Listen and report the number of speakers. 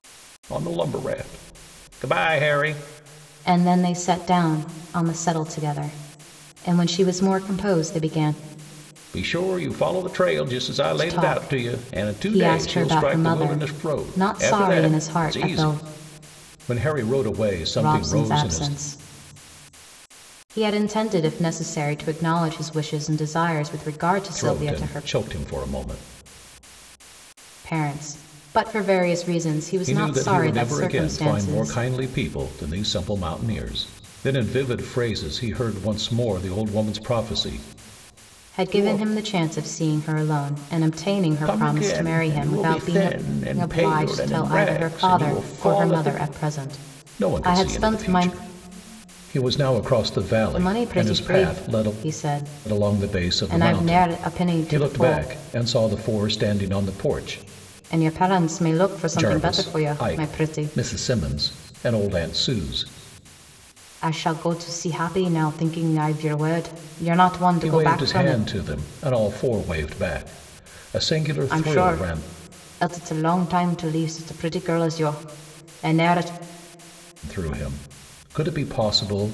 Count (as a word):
two